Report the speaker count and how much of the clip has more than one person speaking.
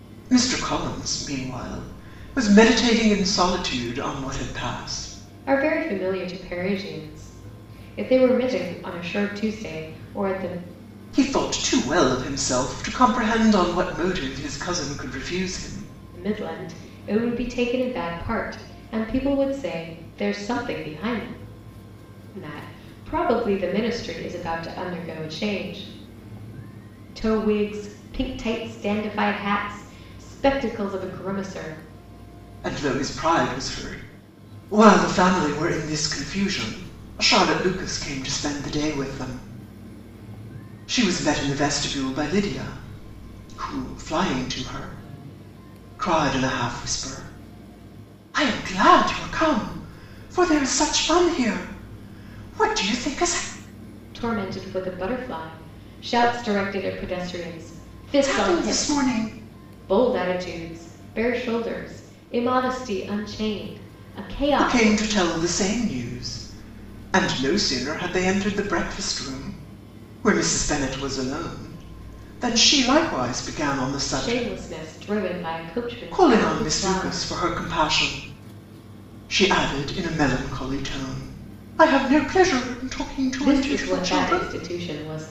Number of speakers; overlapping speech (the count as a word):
two, about 5%